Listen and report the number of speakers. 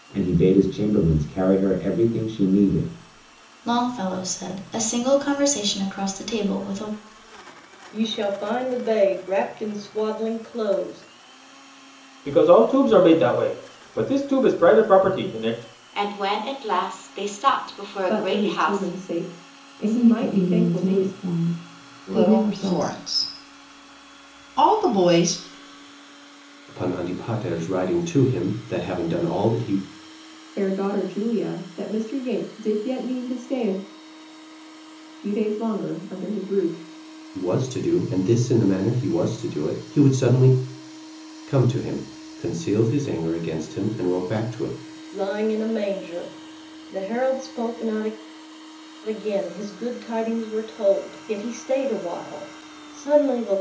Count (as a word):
nine